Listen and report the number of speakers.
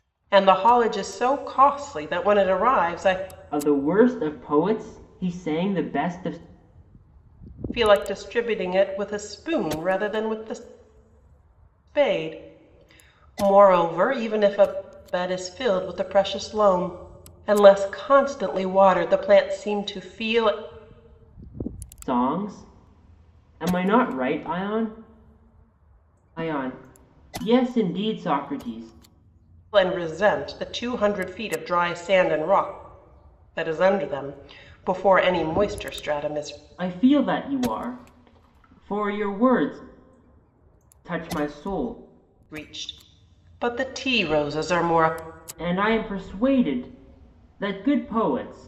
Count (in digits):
2